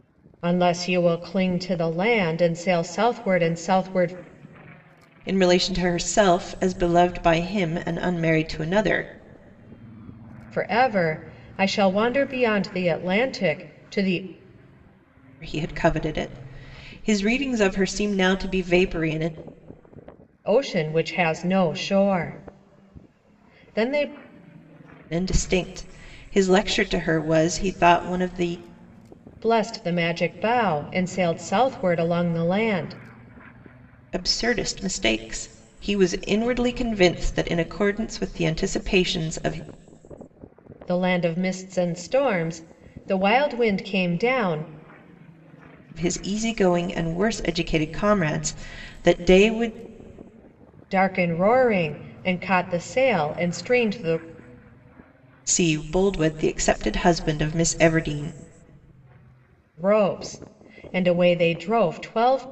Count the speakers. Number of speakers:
2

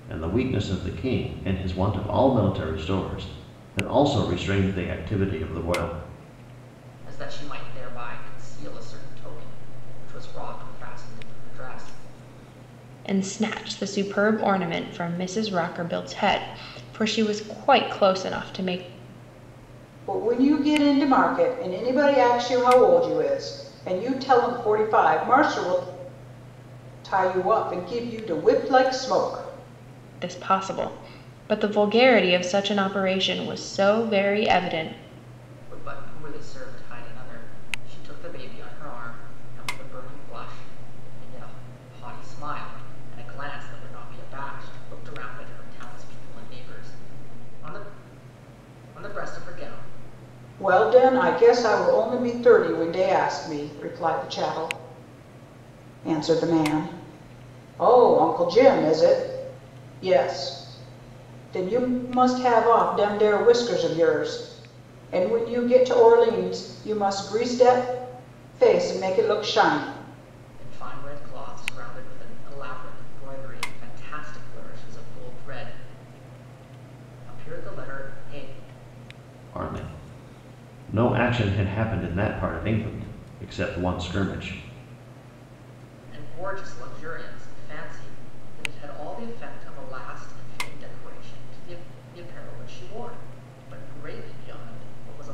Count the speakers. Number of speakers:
4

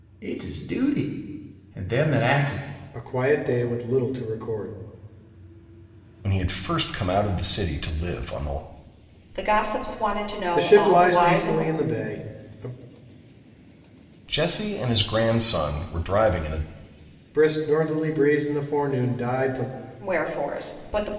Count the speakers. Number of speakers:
4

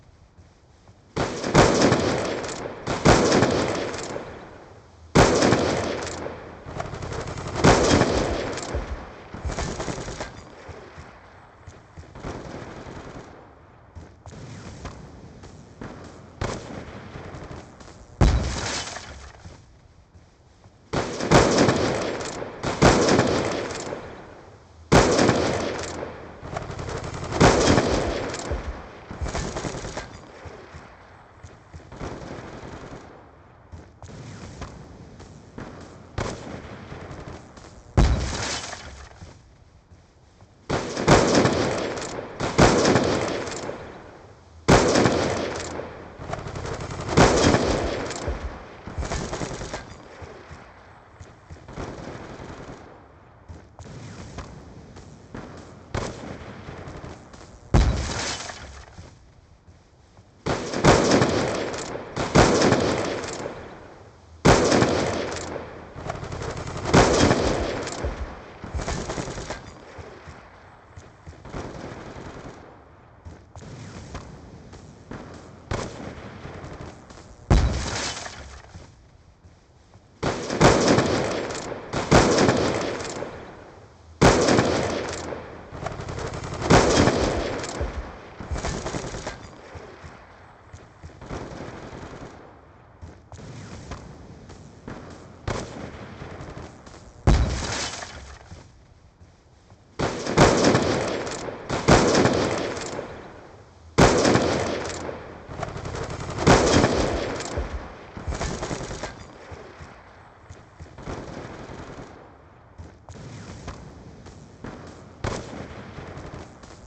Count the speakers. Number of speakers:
0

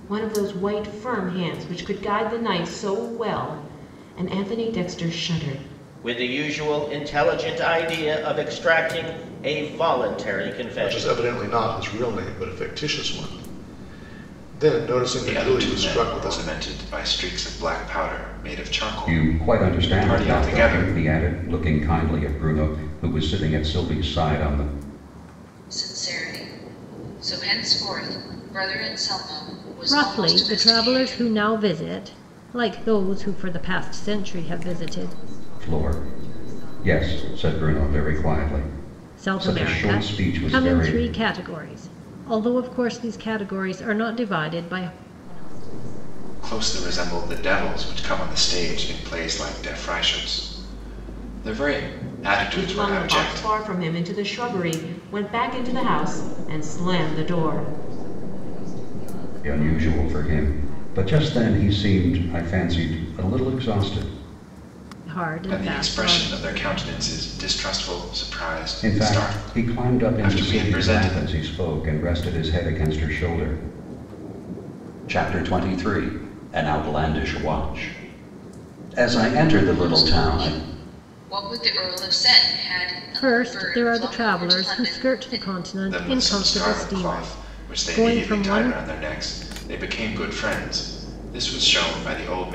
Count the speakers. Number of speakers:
8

